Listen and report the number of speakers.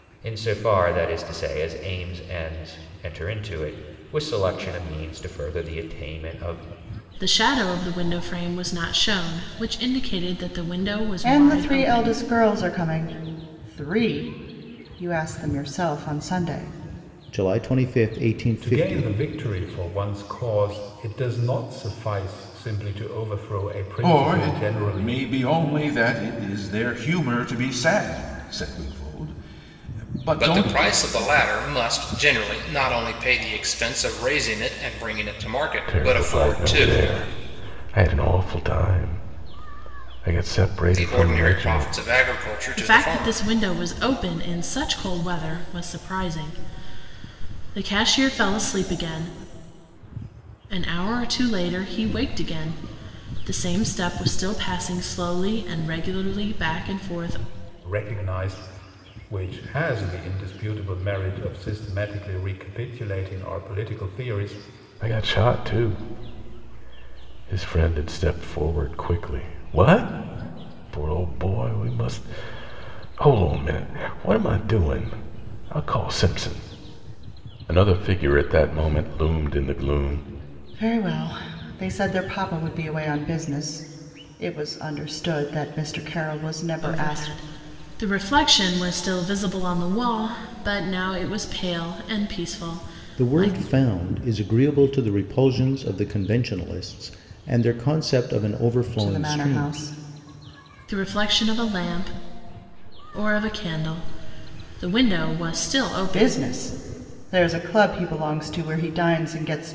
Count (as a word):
eight